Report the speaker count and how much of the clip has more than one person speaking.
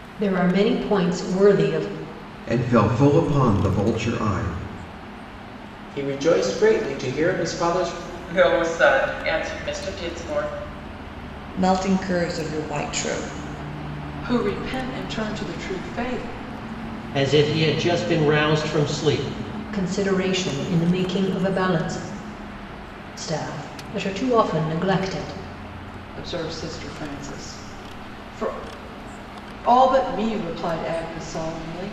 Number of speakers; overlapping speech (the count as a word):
seven, no overlap